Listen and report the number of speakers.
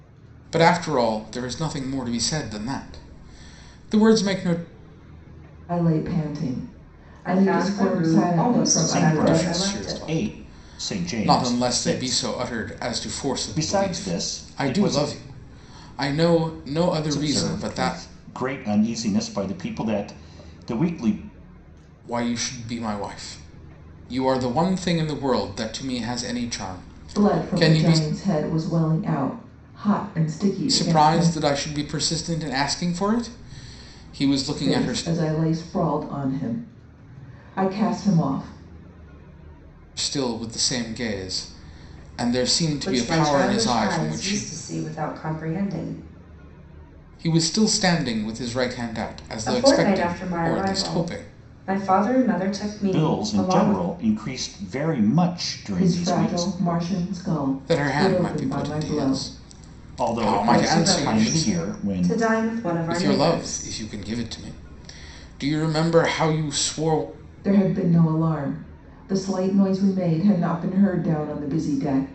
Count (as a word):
four